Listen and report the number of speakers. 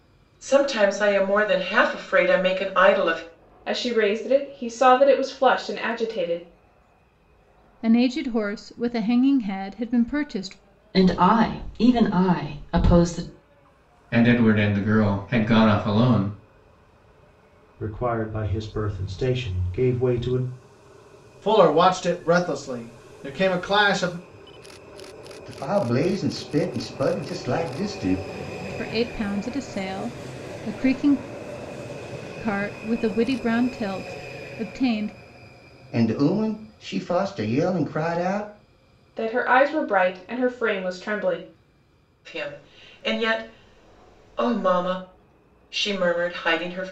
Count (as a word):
eight